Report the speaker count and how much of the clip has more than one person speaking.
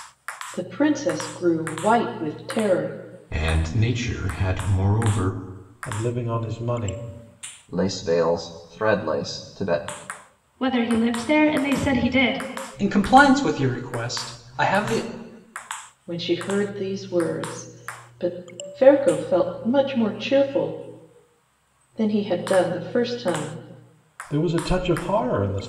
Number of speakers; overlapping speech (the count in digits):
6, no overlap